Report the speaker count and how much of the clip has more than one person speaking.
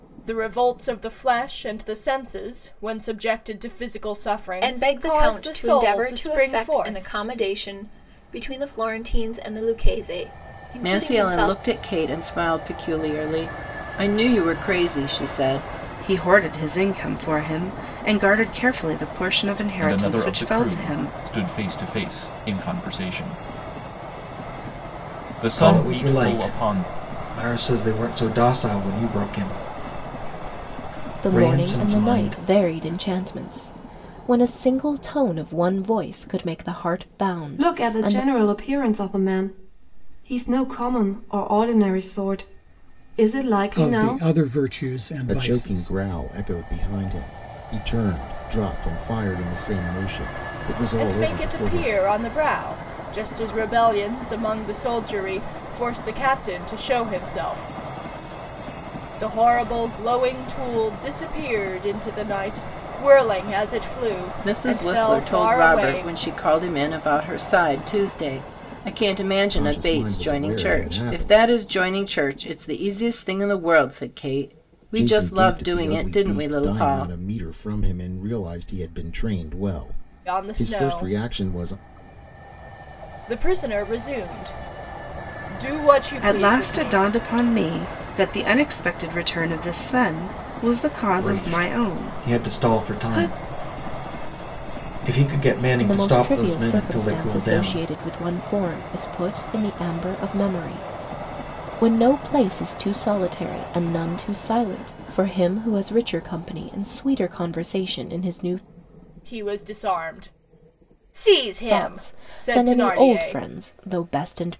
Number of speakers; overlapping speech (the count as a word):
ten, about 21%